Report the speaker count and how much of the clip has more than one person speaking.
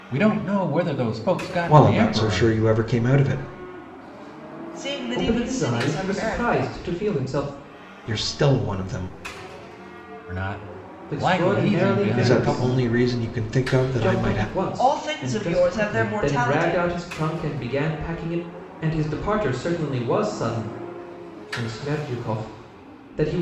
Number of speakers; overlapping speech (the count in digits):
4, about 31%